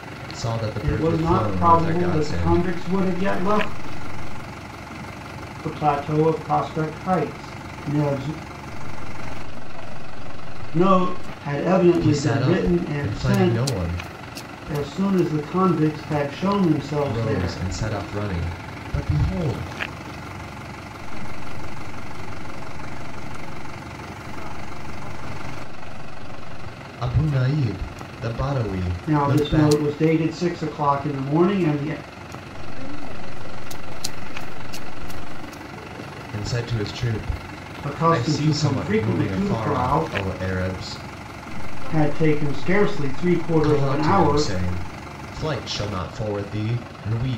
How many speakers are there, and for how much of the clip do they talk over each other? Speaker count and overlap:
three, about 25%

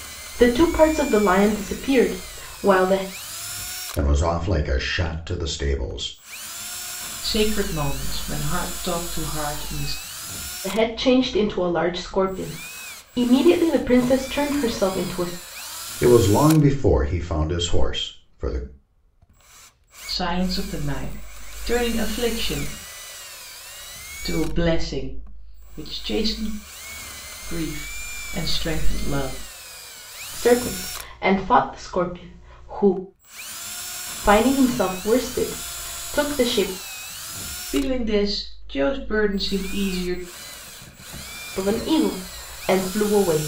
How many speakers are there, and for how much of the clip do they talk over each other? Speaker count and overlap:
three, no overlap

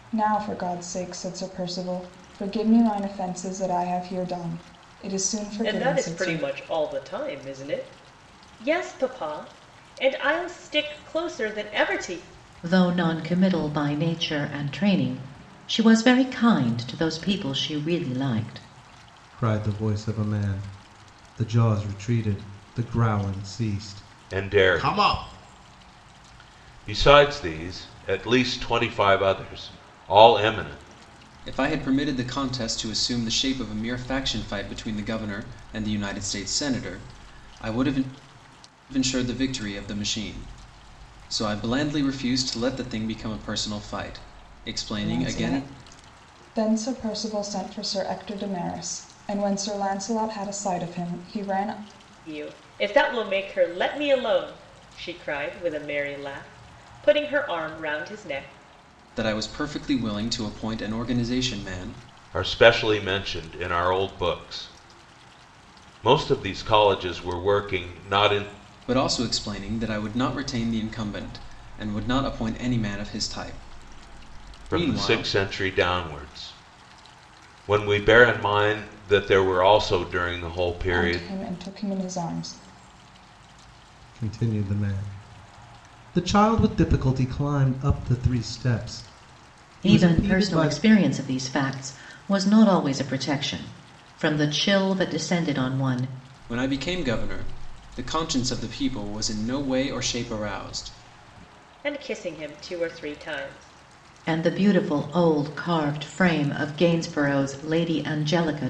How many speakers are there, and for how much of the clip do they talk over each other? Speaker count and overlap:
six, about 4%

